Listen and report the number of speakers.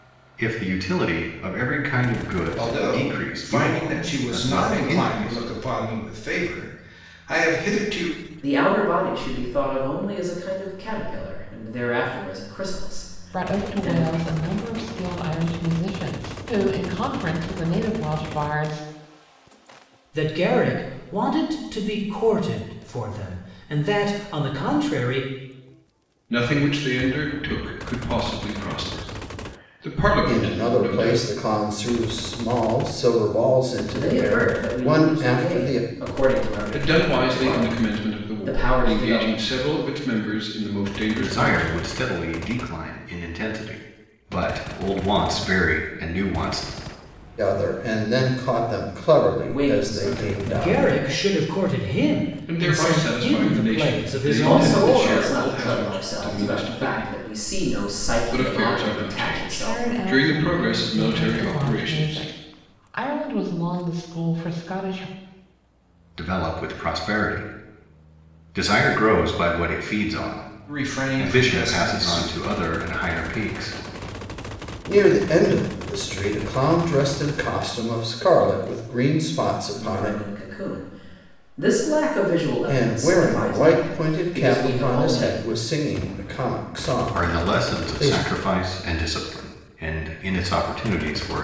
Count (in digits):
7